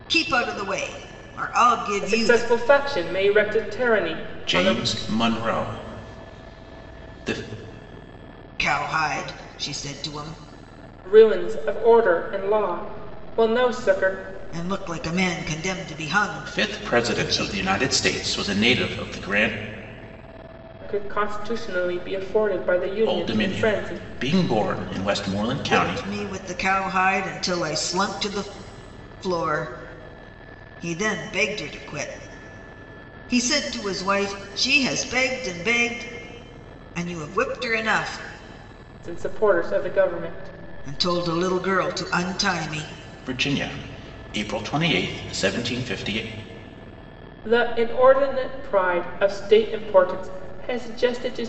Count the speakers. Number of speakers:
3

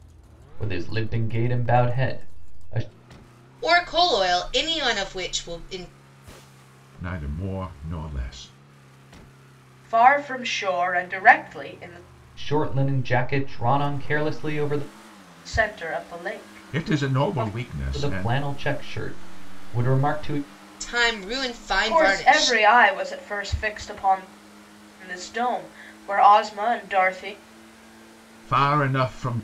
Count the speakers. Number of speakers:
4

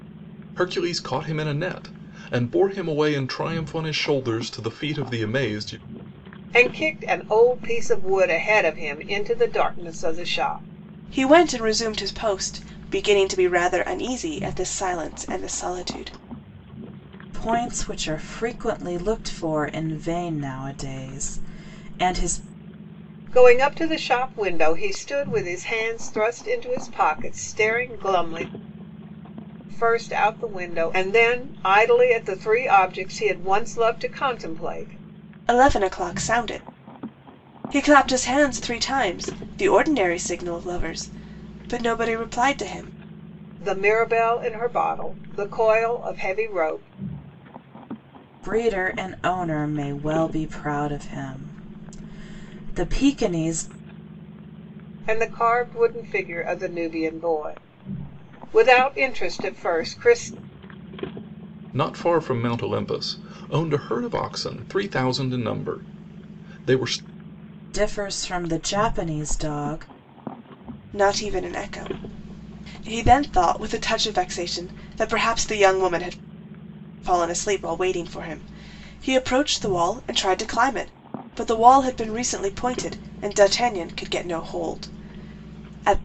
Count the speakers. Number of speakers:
4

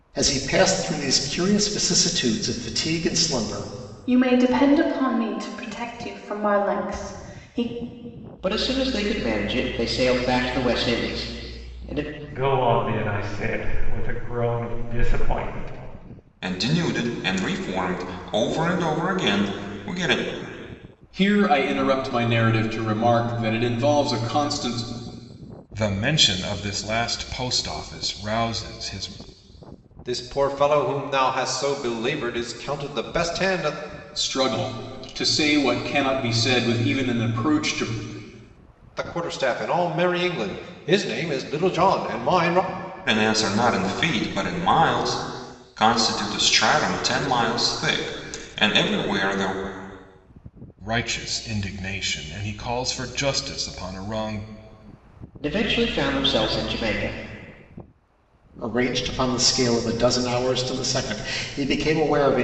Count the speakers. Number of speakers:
8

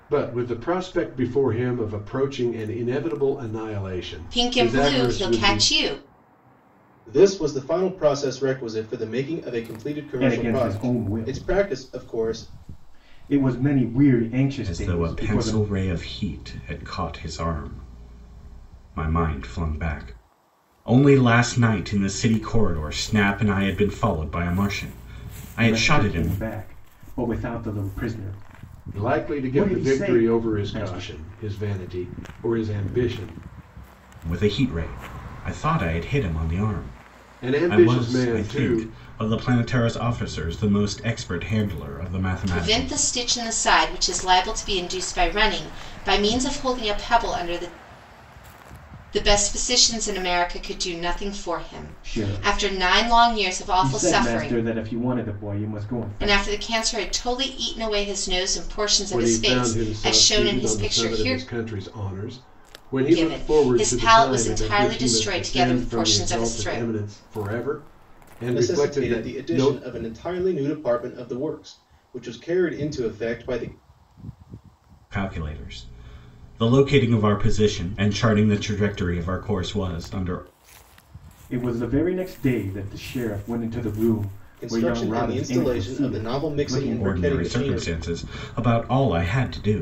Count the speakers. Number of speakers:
5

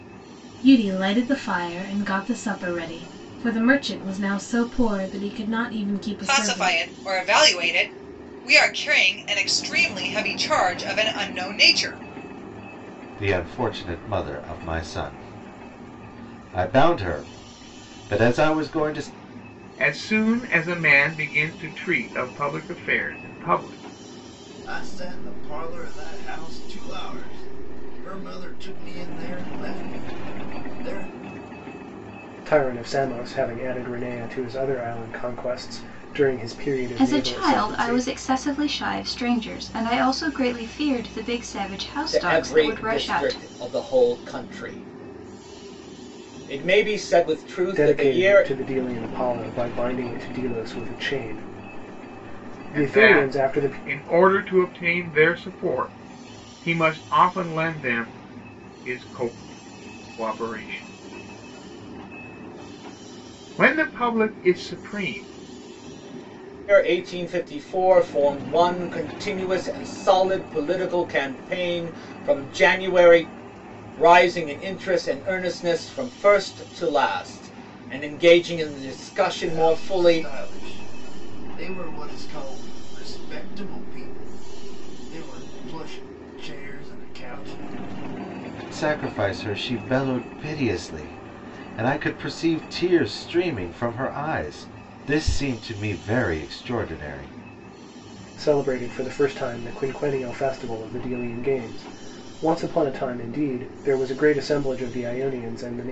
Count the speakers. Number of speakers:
8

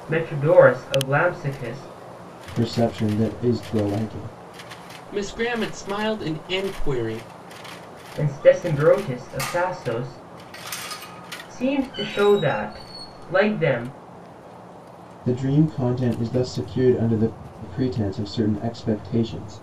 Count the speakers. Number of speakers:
3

